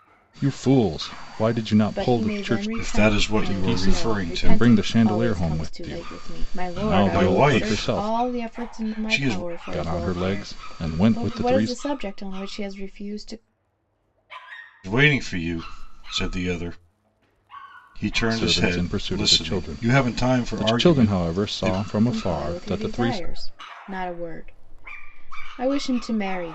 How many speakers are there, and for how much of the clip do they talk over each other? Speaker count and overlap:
three, about 54%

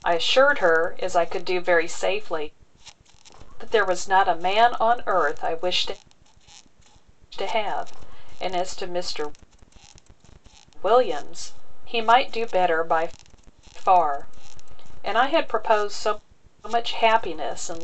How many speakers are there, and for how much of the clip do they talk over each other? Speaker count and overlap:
one, no overlap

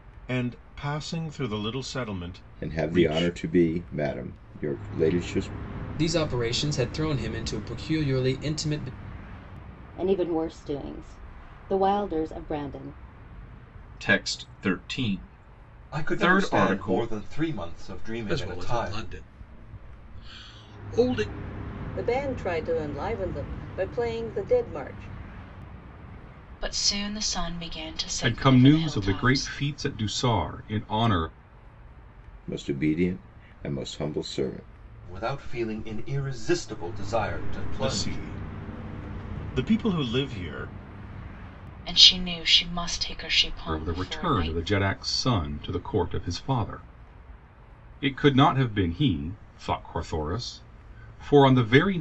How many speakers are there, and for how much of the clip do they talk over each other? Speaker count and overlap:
ten, about 11%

